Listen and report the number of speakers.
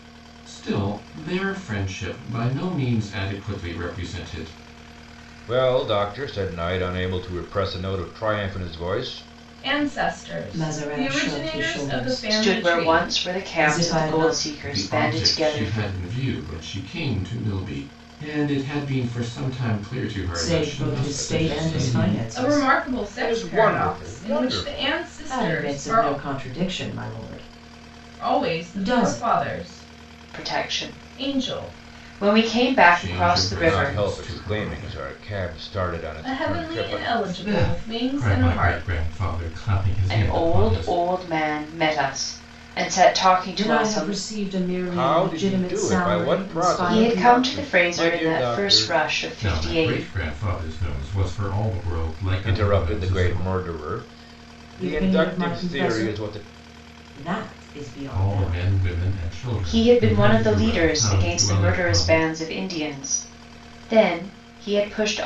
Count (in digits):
5